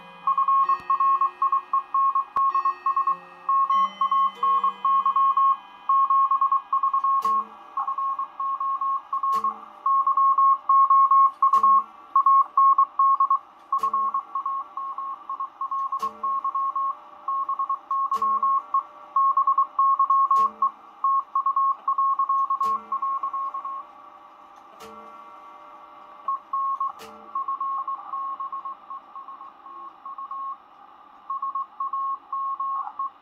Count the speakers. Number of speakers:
0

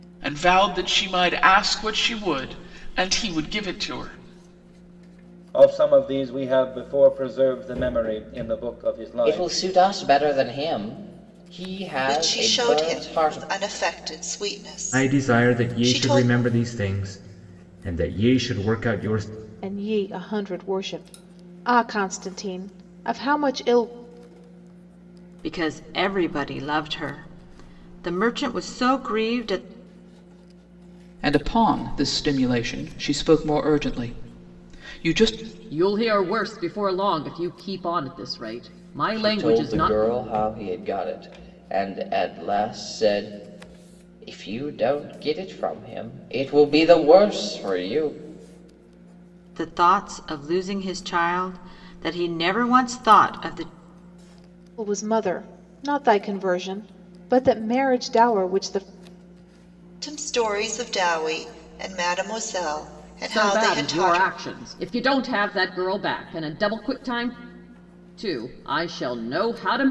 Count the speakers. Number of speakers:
9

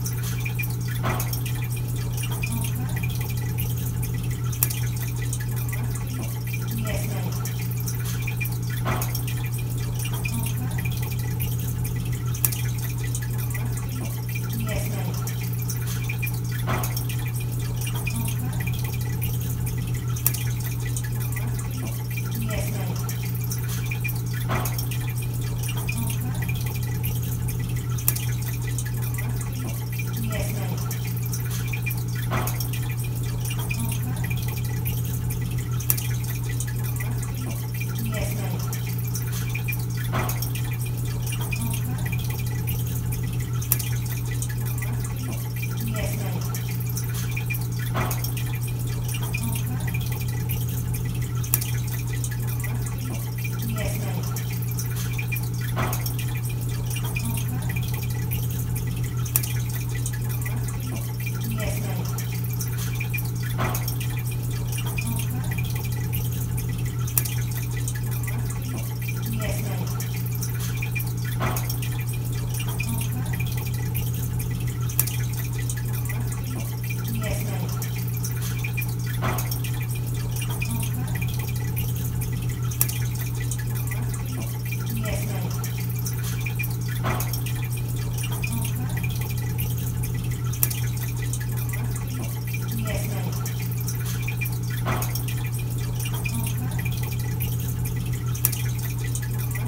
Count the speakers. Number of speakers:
0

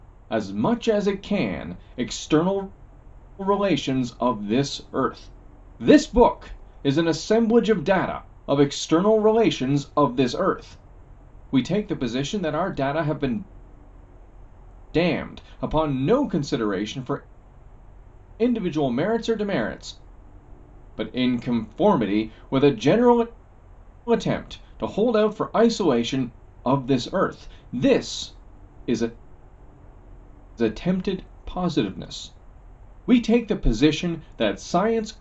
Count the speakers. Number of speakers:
1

